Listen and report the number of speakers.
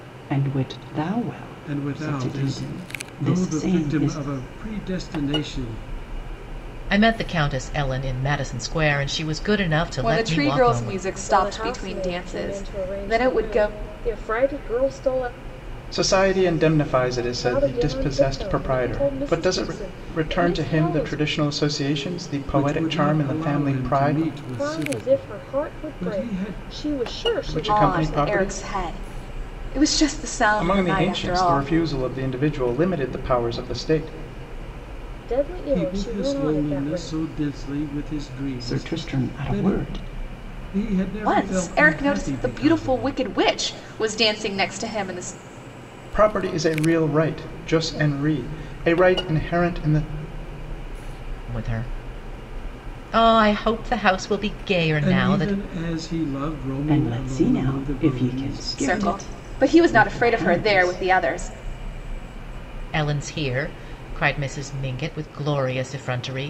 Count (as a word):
six